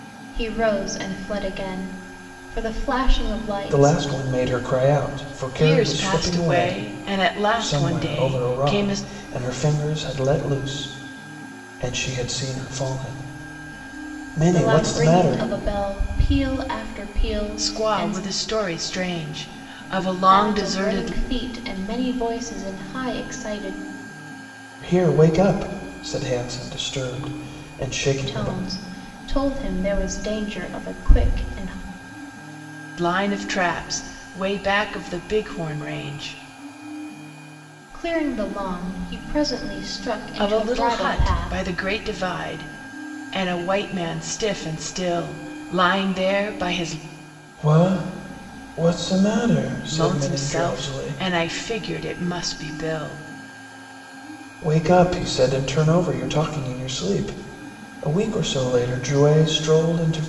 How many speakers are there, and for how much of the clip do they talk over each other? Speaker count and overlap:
three, about 14%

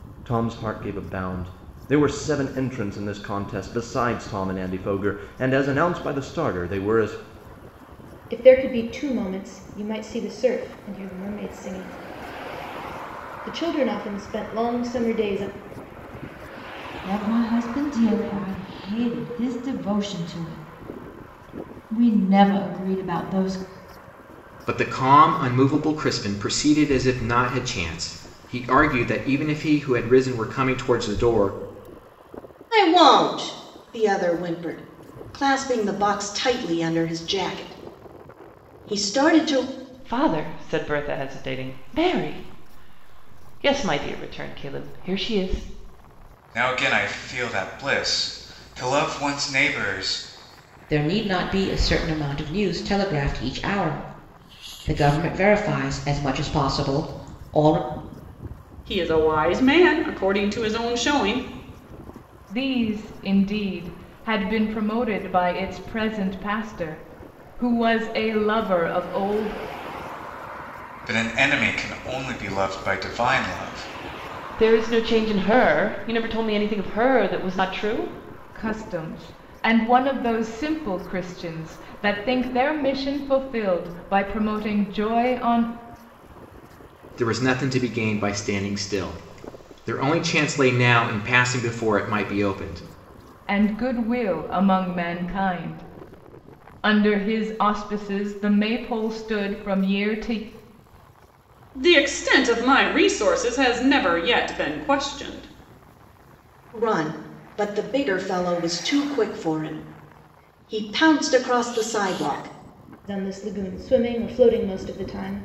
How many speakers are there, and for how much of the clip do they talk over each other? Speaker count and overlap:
ten, no overlap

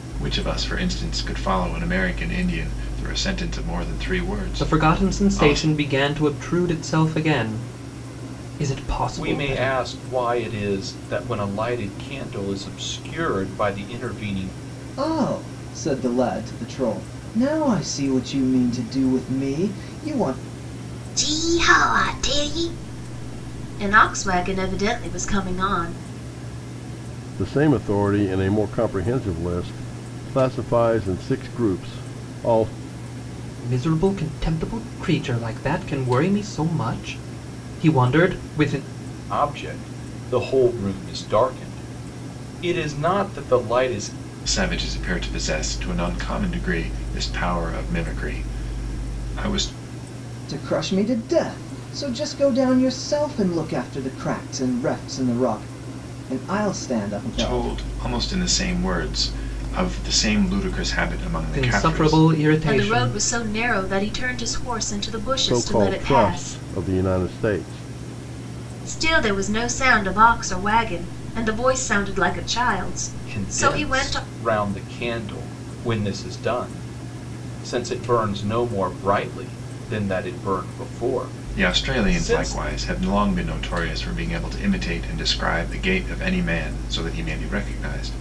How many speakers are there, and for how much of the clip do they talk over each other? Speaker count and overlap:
six, about 8%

